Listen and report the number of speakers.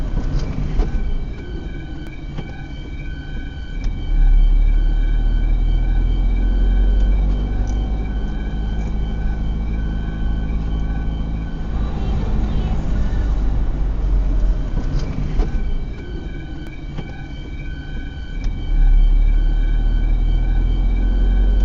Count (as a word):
zero